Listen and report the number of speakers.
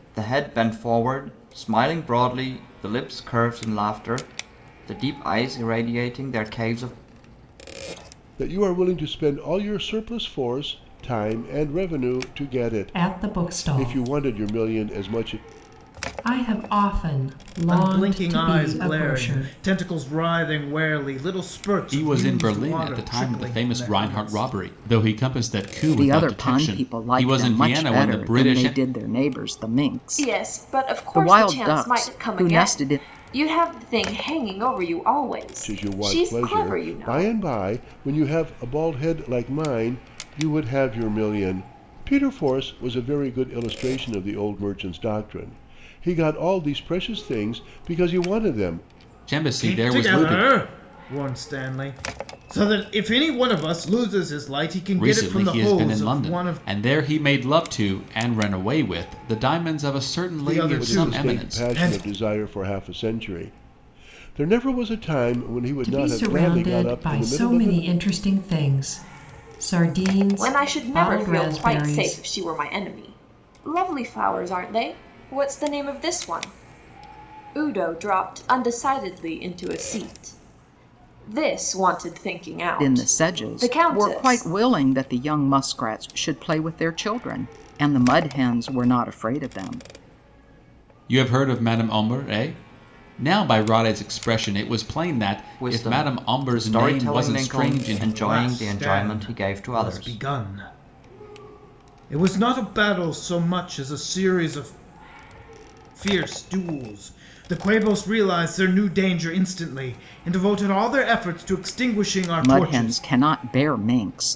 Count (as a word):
seven